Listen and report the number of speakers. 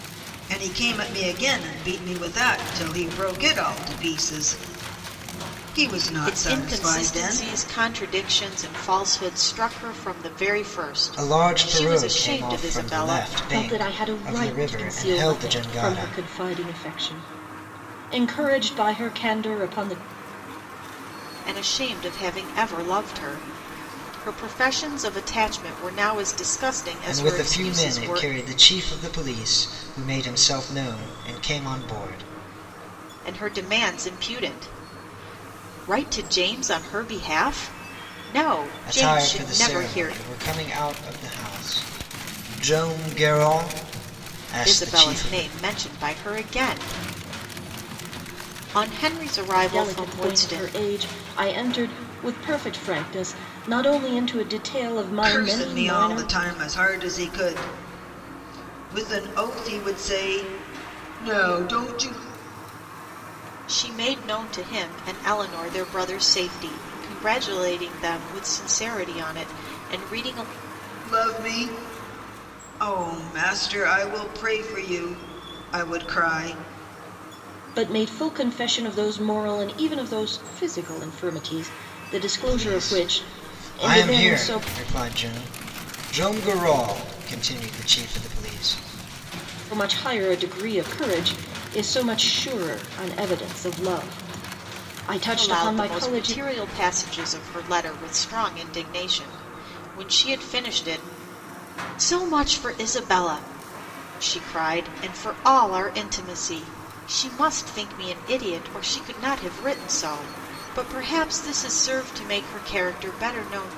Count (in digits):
4